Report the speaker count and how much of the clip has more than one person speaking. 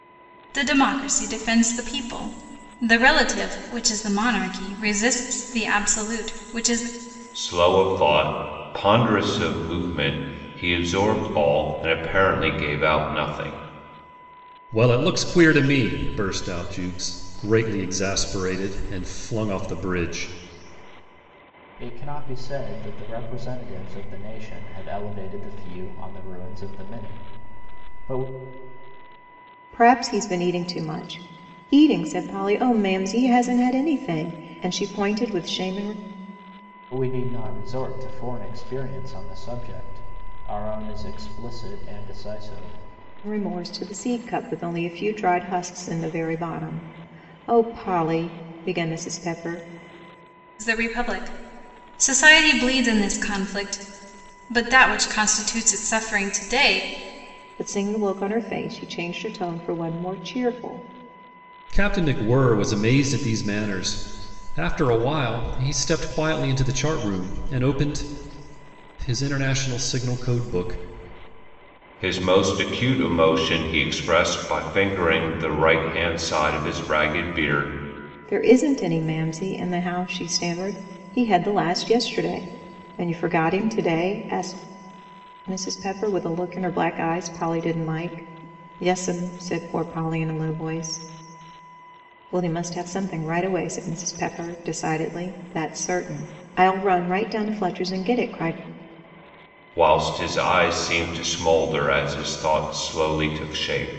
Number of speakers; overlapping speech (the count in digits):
5, no overlap